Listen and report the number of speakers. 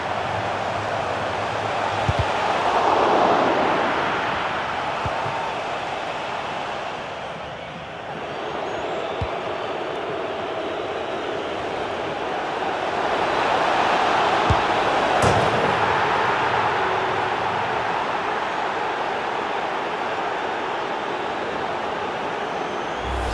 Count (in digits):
0